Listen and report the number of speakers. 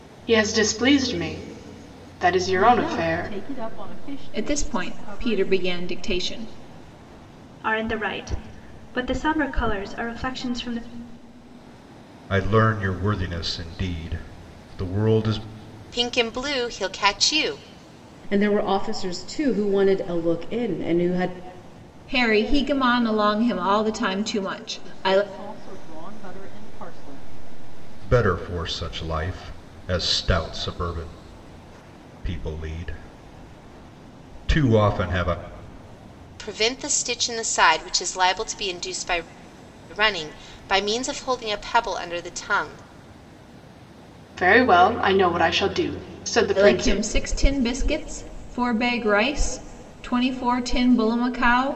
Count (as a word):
seven